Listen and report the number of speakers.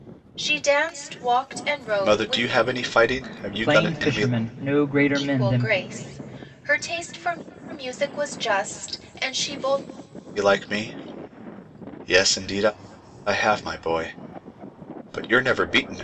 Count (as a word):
three